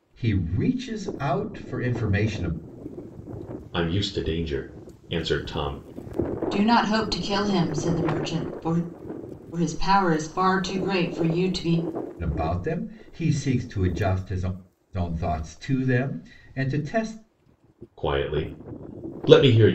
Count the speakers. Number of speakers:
3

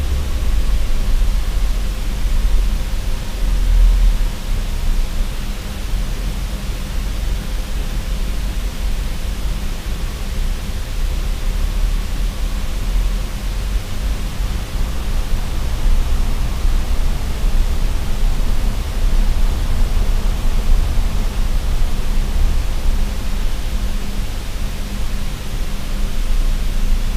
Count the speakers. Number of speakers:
0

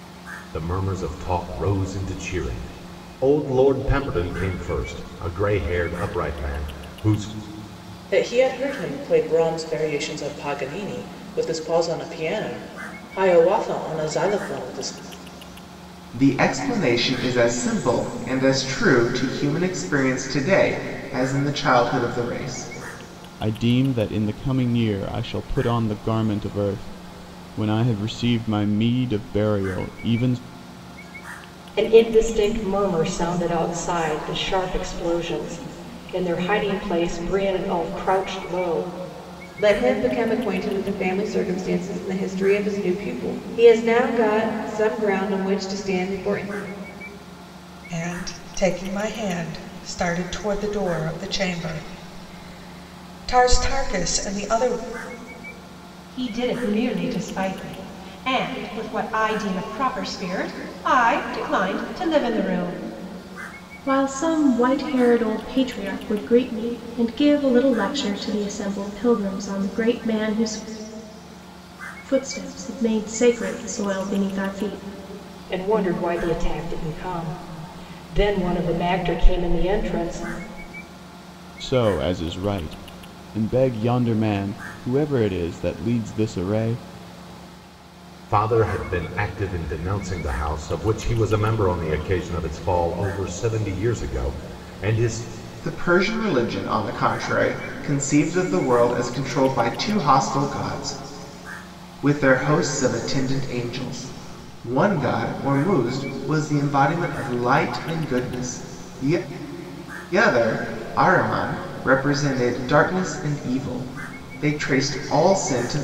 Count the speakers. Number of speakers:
9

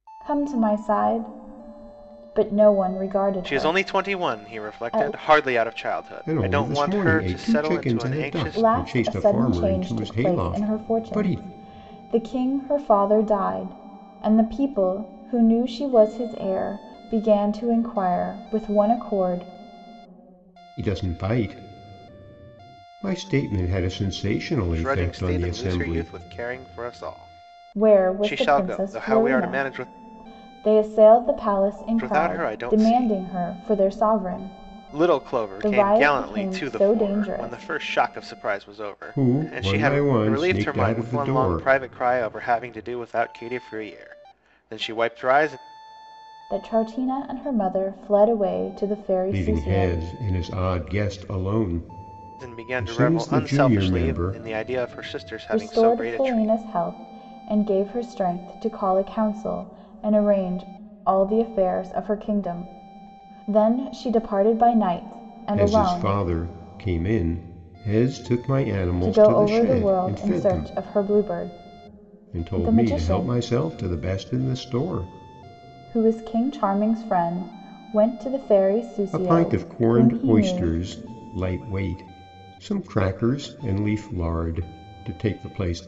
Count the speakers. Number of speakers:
3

